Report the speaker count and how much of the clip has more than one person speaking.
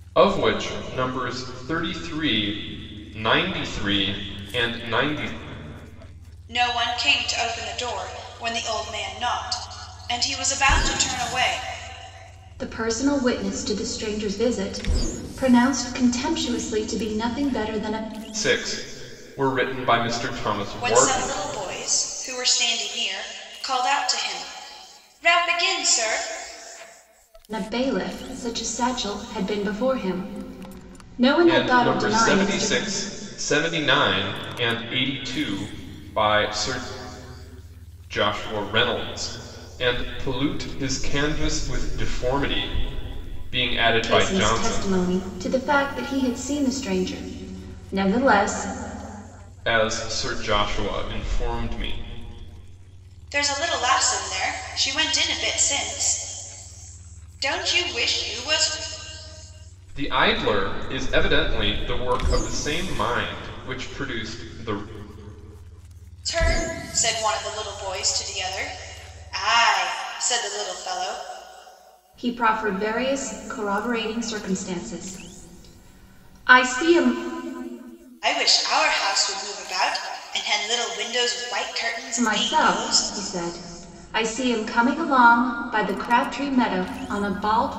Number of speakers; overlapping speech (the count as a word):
three, about 4%